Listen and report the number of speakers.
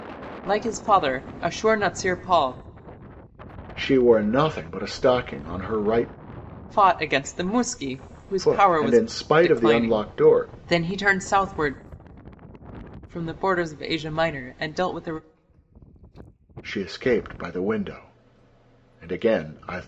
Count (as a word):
two